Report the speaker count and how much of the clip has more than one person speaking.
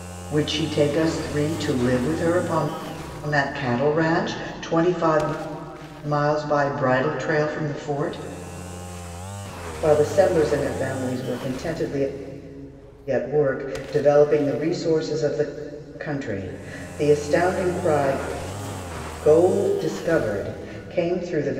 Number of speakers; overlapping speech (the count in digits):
1, no overlap